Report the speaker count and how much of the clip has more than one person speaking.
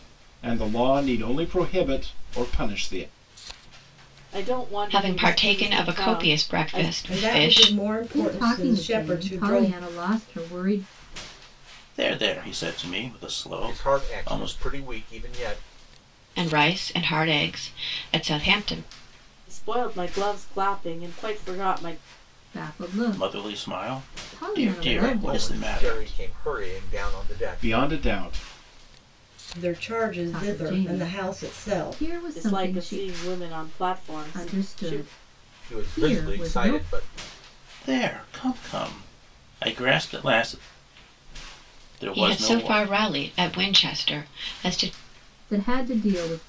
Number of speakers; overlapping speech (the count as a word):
seven, about 33%